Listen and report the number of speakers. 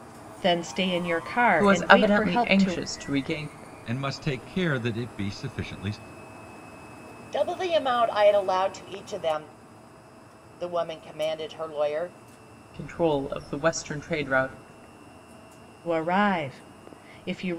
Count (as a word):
four